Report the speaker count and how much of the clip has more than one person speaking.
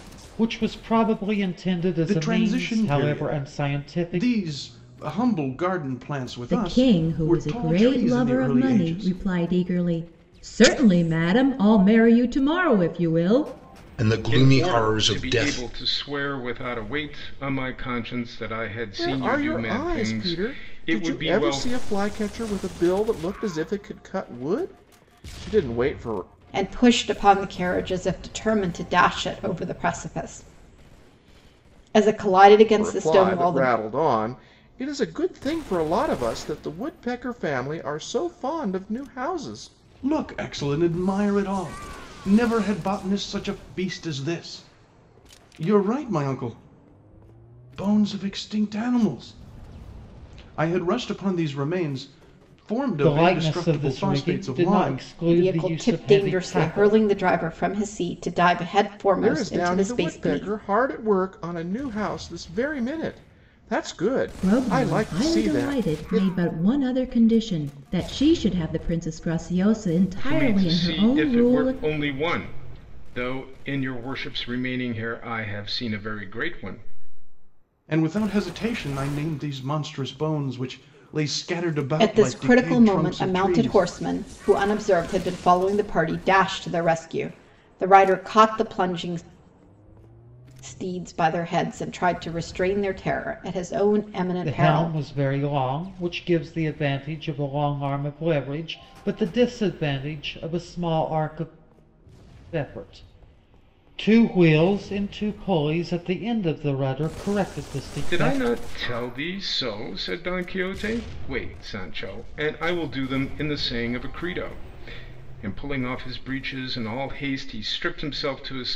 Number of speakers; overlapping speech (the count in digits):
7, about 19%